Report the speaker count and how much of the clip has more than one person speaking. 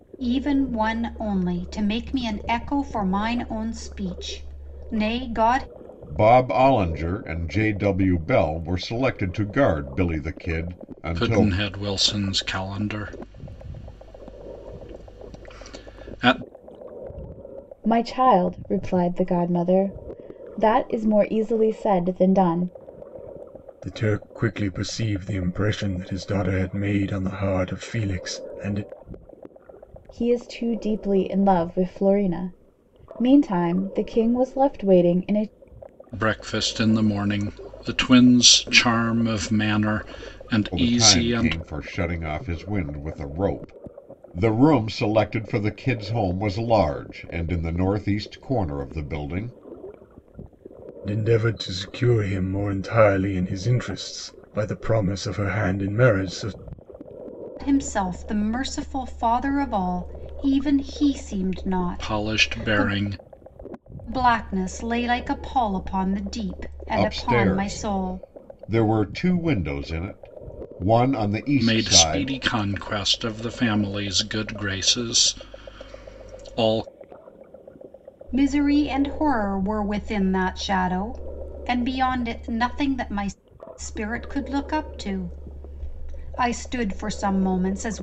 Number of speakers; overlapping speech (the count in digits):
5, about 5%